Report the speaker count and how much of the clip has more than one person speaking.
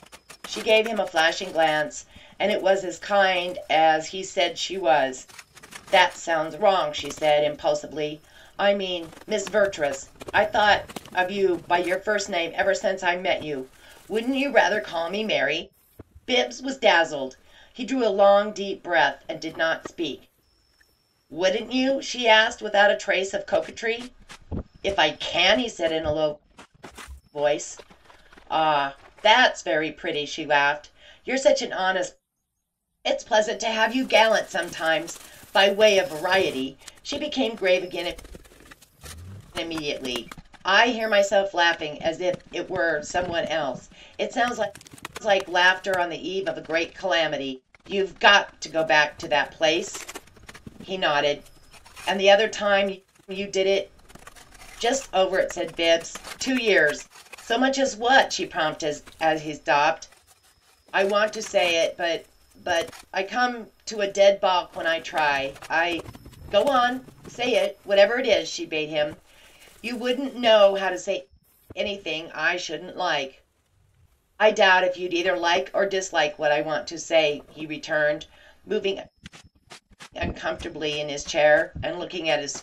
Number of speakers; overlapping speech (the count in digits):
1, no overlap